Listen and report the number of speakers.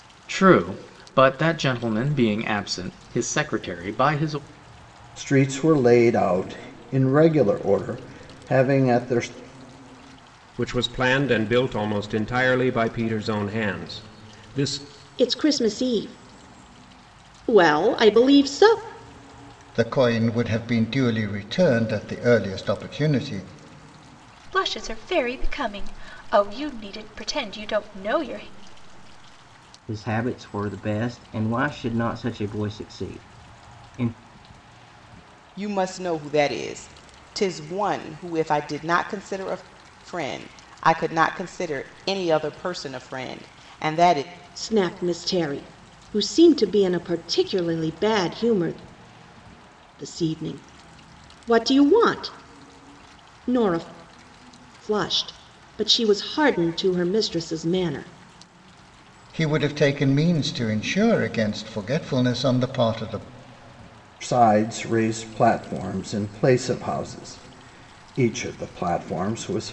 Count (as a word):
eight